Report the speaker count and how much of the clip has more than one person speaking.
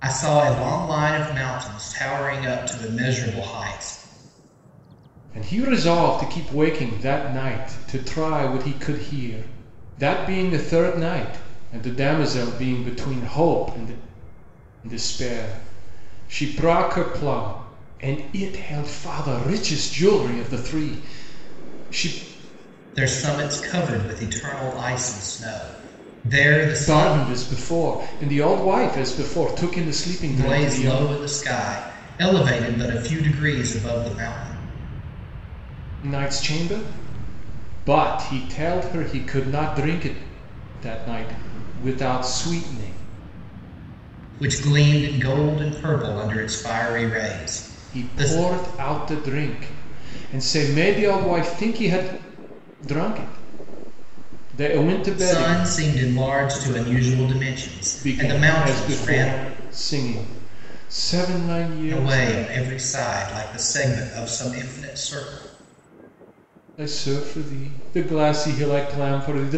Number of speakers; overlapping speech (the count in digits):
2, about 6%